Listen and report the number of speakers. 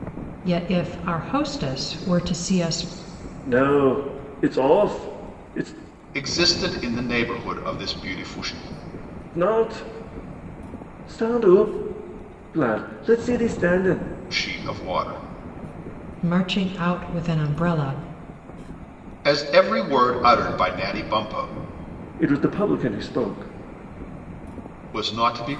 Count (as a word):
three